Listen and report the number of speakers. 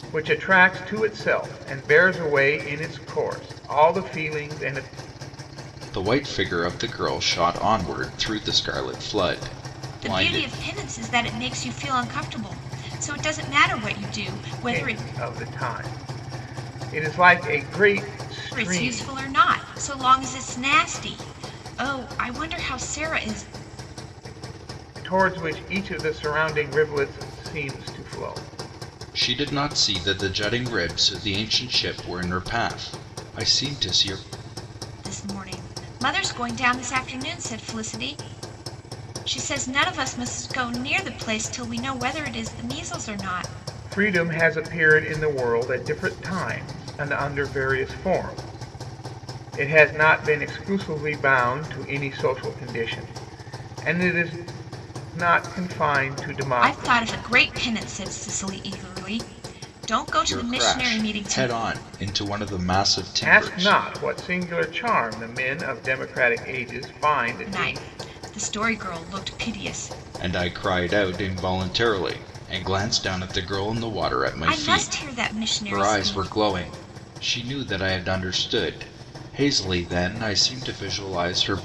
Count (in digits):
3